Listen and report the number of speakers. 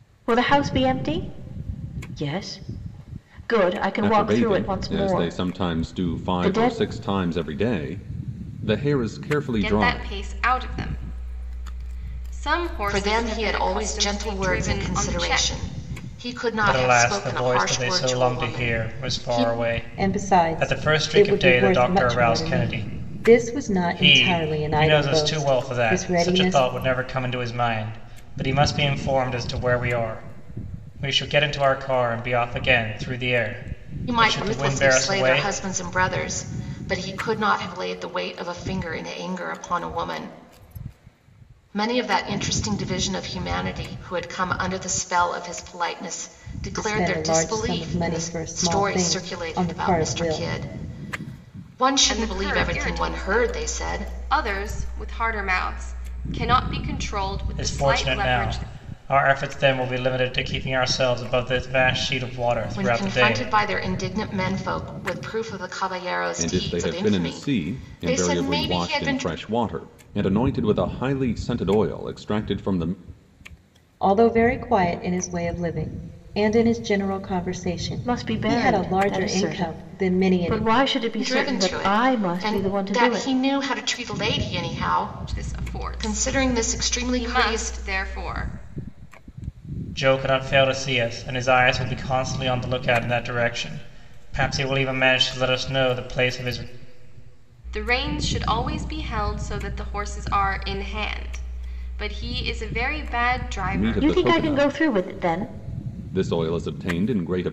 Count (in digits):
6